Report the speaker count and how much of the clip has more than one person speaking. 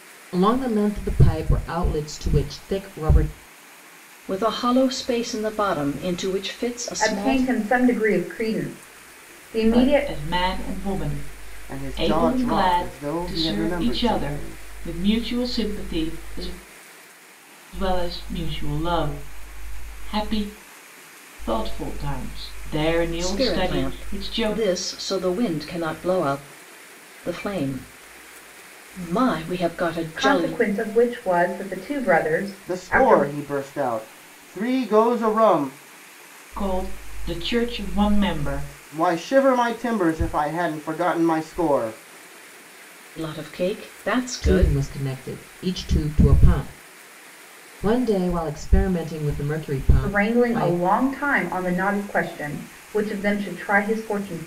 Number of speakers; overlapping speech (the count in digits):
5, about 13%